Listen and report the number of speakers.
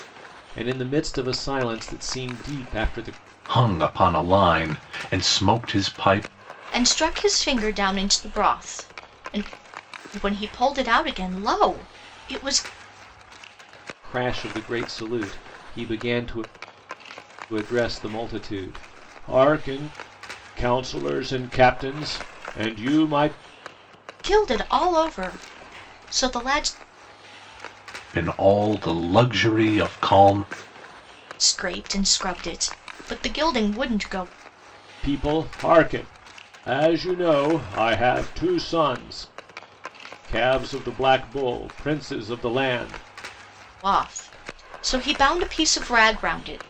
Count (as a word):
three